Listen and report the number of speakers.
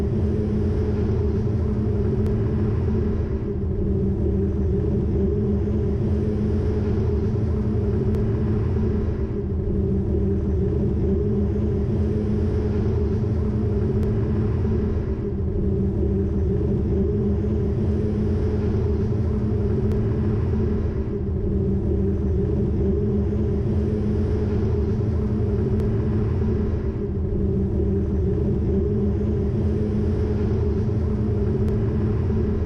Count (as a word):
zero